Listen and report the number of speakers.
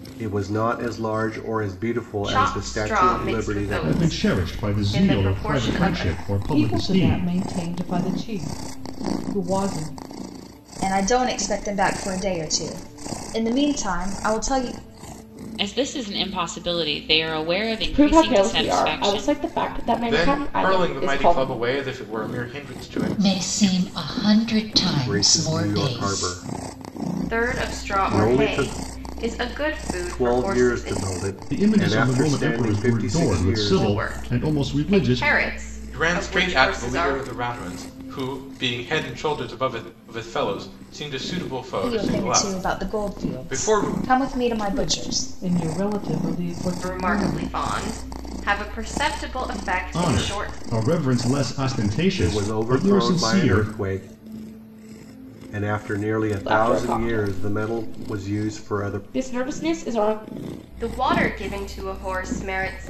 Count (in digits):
9